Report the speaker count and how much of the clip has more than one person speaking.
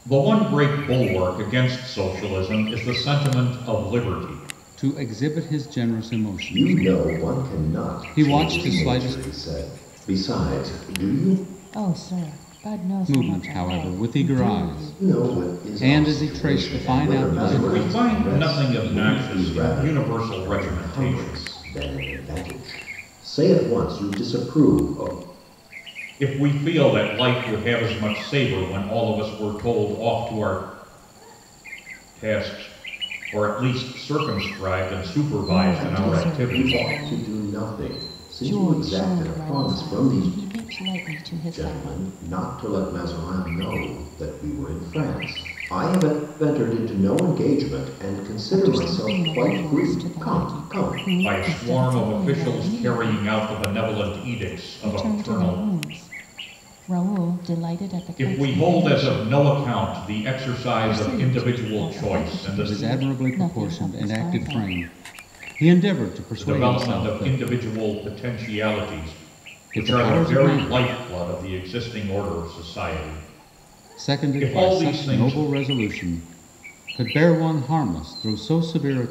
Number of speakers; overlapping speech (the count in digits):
4, about 37%